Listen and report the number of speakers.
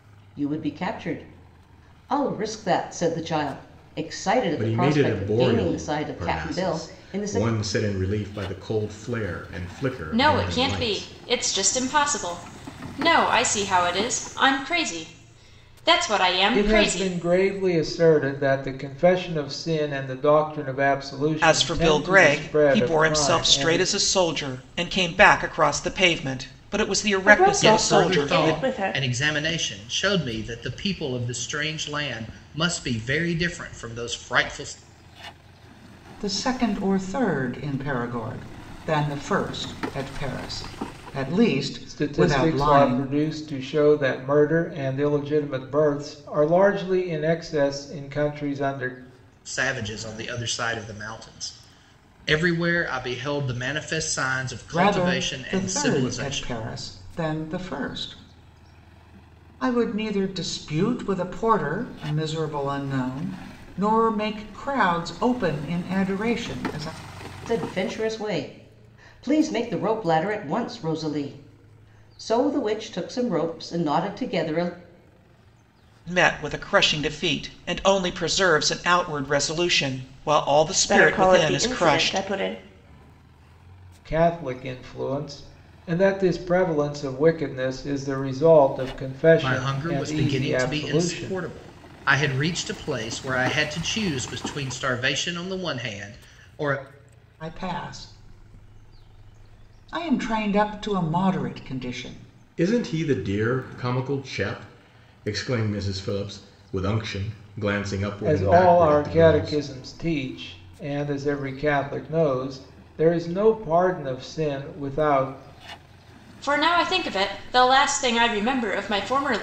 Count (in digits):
8